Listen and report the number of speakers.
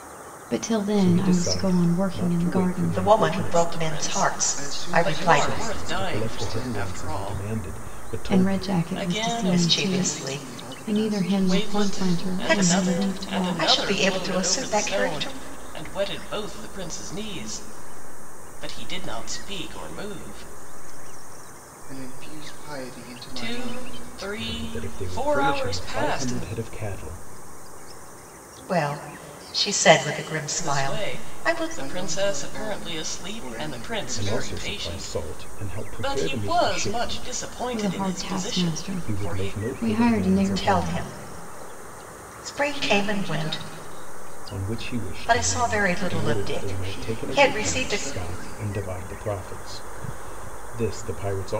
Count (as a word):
five